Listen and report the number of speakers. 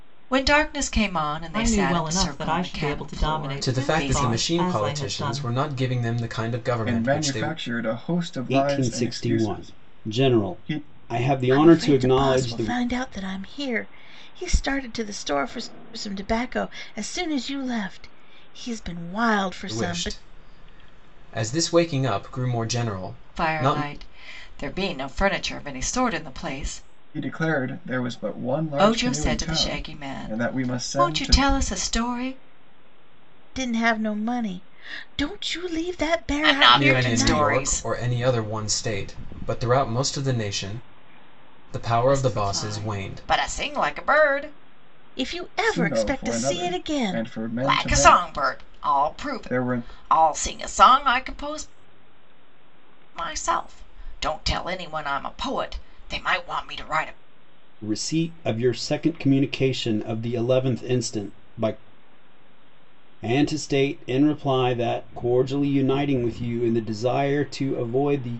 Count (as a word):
six